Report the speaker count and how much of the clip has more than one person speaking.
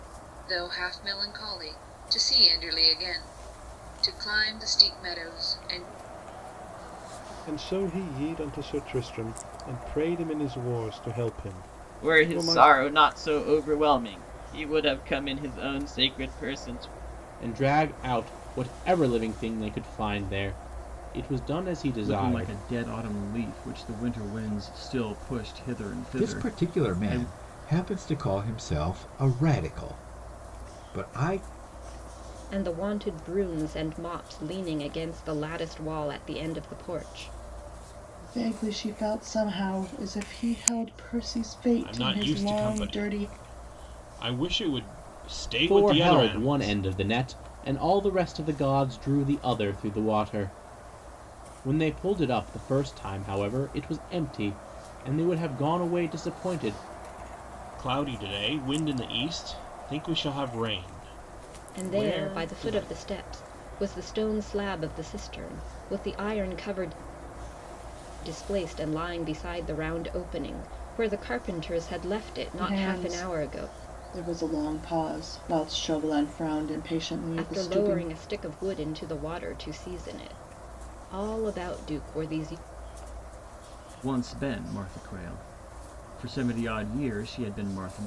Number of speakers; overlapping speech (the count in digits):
9, about 9%